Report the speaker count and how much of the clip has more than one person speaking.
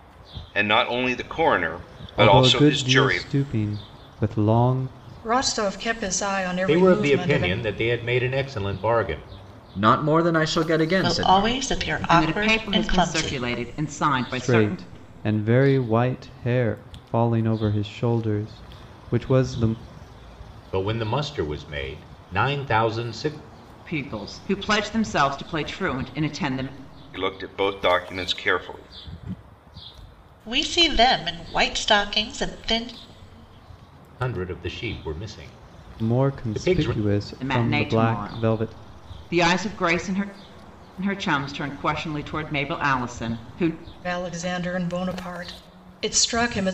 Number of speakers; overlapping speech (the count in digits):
7, about 15%